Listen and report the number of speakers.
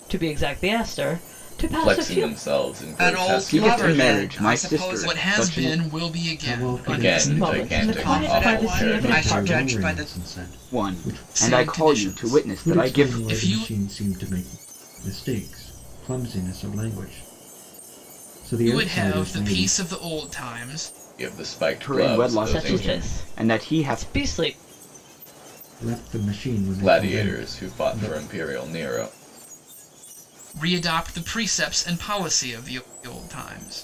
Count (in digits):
6